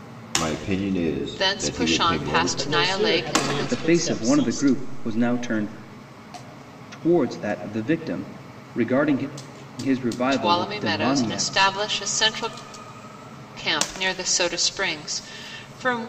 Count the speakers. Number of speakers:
4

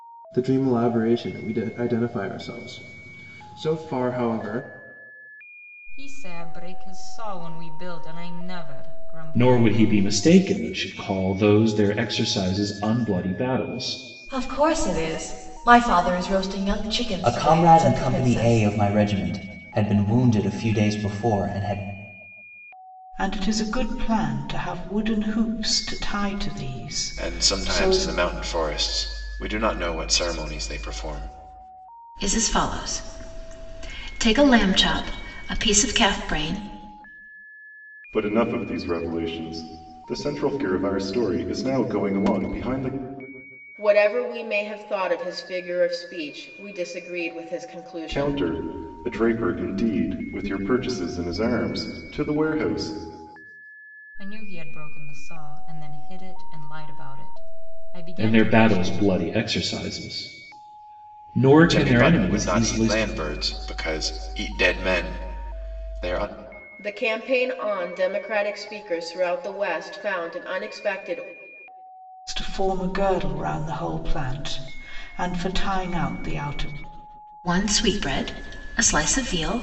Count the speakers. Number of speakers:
10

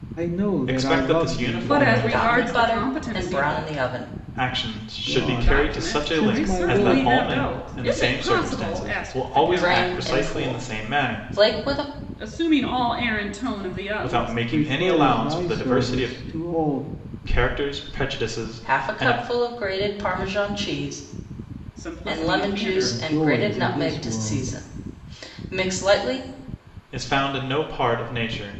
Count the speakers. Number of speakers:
4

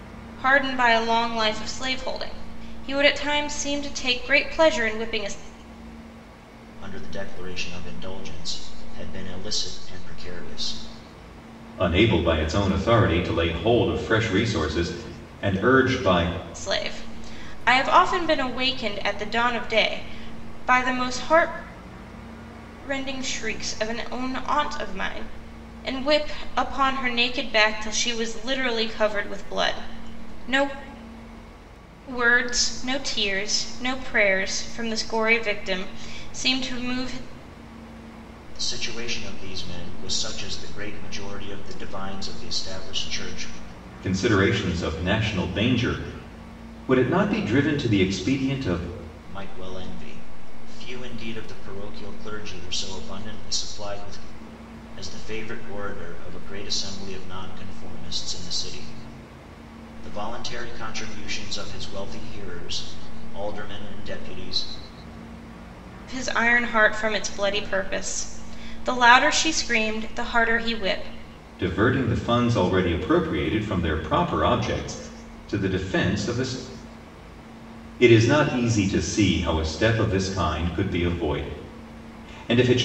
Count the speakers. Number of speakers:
3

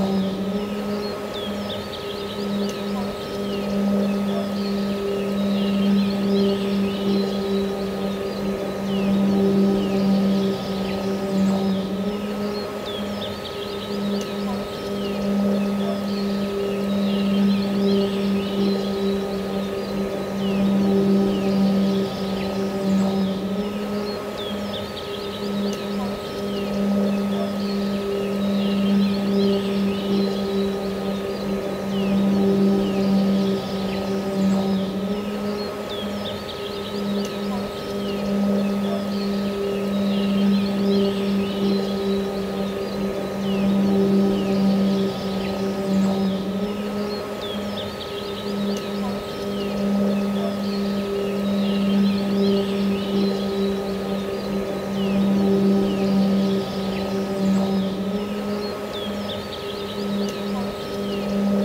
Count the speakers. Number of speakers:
0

